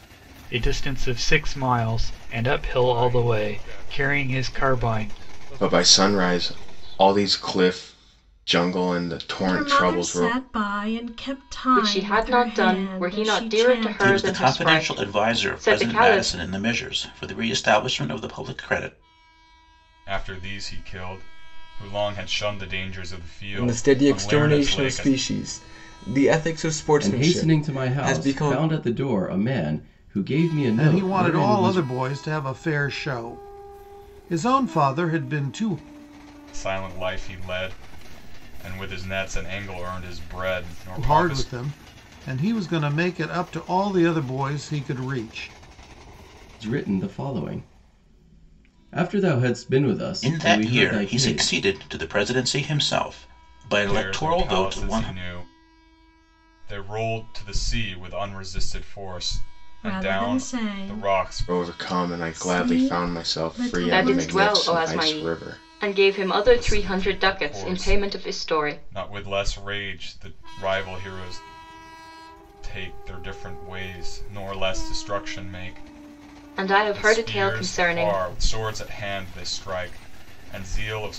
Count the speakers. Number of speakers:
ten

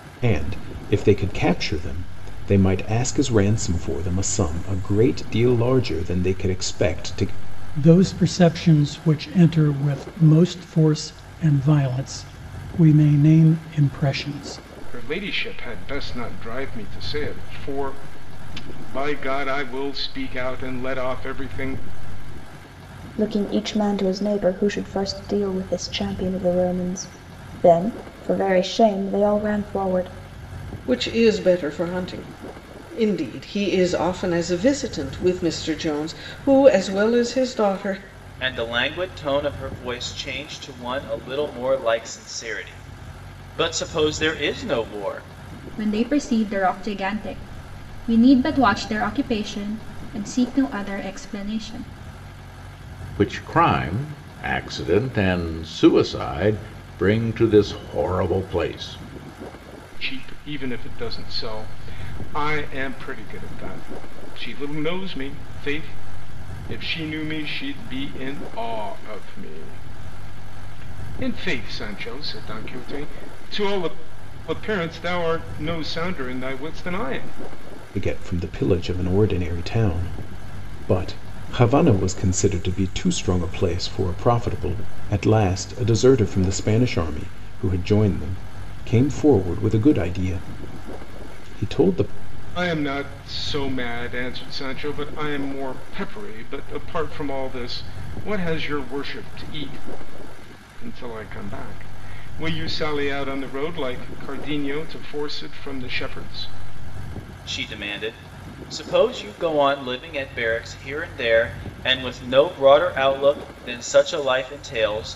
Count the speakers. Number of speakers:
eight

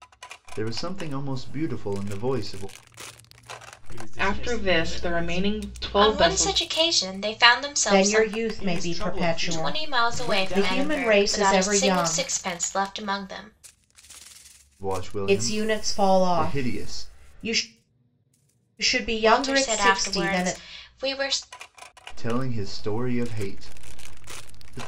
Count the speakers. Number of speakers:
five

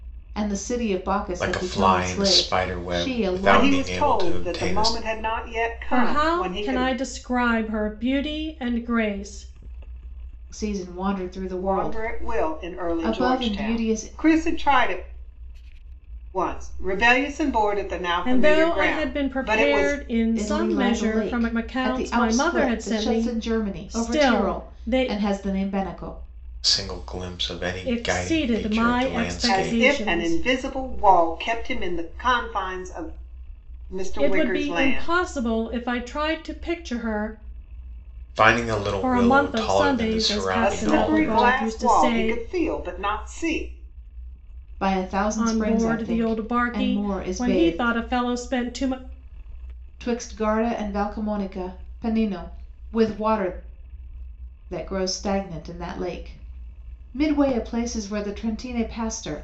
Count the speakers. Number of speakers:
four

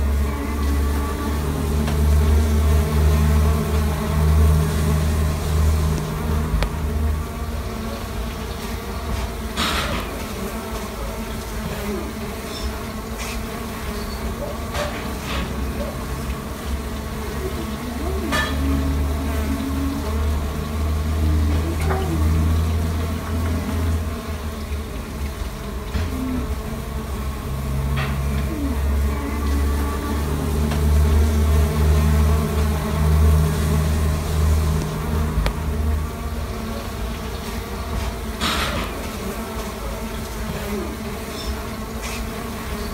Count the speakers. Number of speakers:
zero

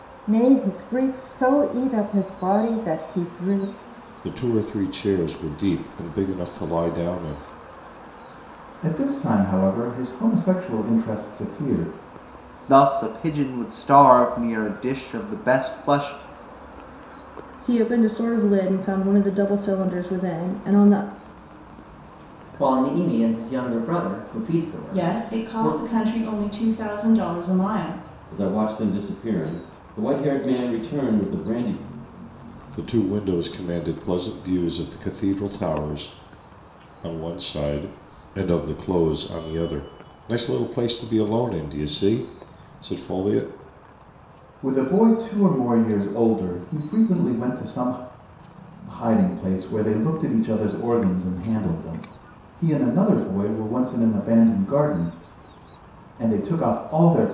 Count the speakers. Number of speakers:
eight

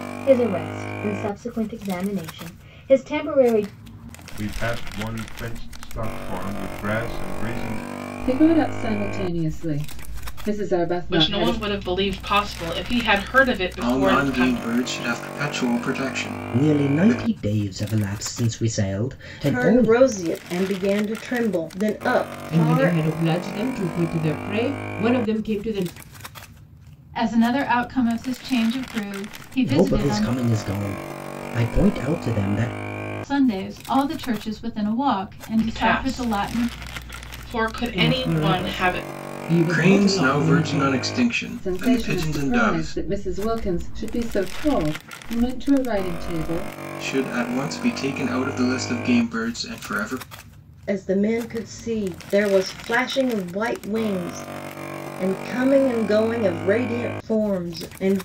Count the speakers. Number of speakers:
nine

